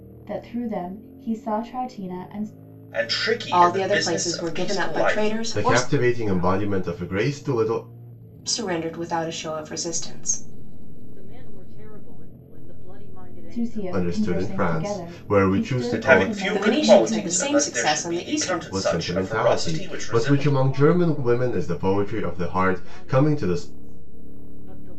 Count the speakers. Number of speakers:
five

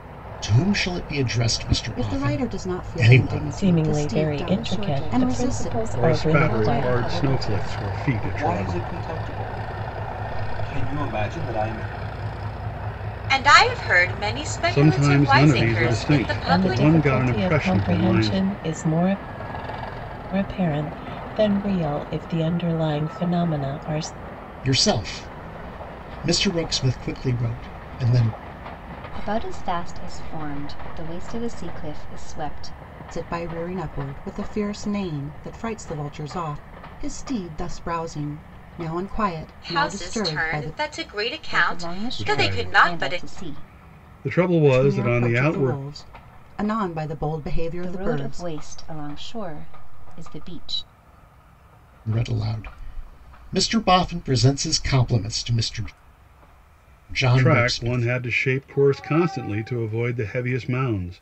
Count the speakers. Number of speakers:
seven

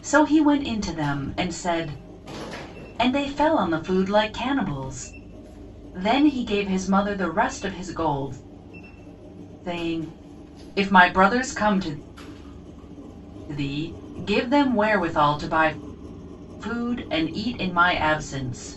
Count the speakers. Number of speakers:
one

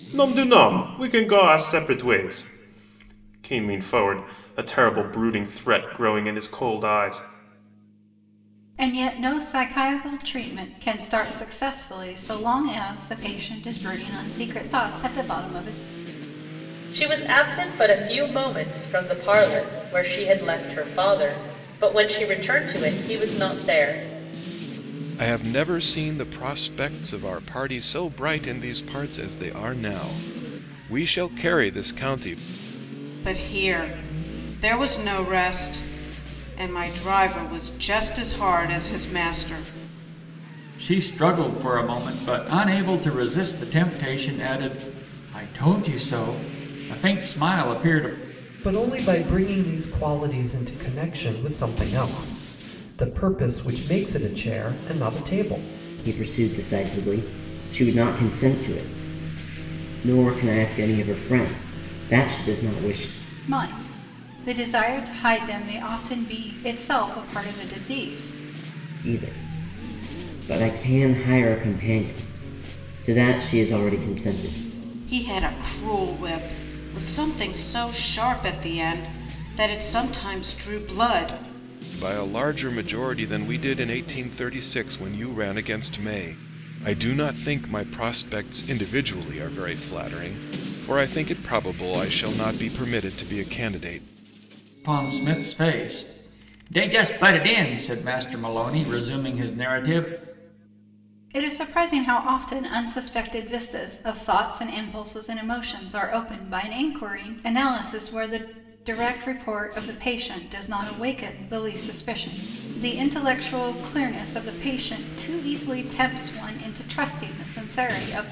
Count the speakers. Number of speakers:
eight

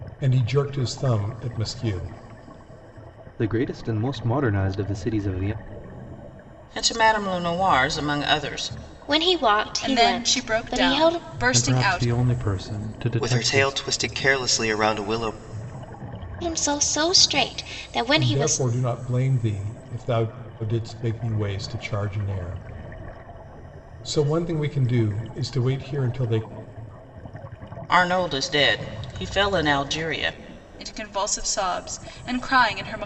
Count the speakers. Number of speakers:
seven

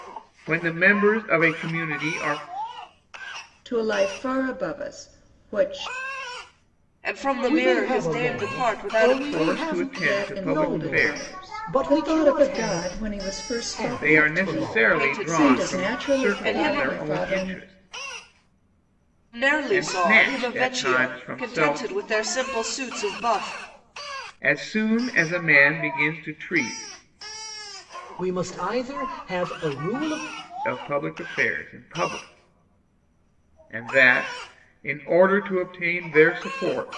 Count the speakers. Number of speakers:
four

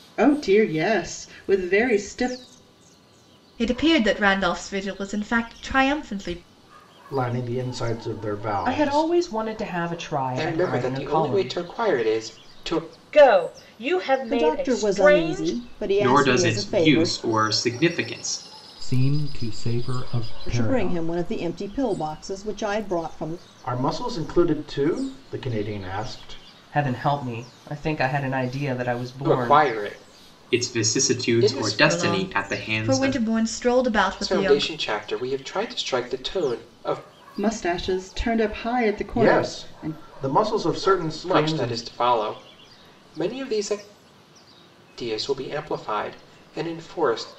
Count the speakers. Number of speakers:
nine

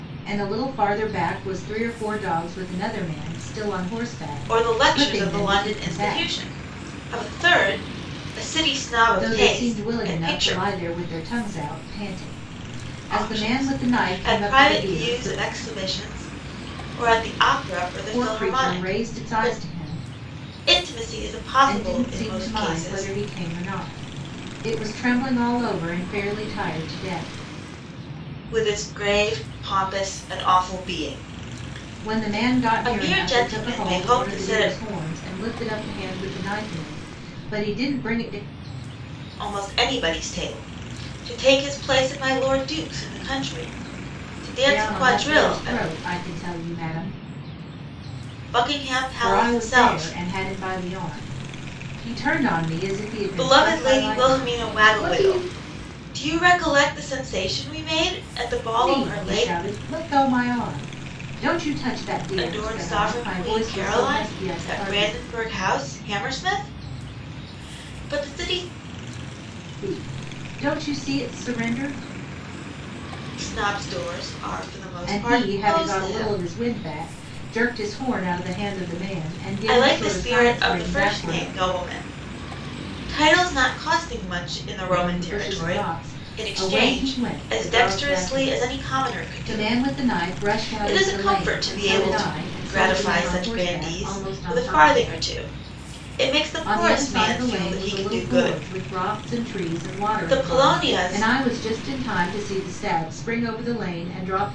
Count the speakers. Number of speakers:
two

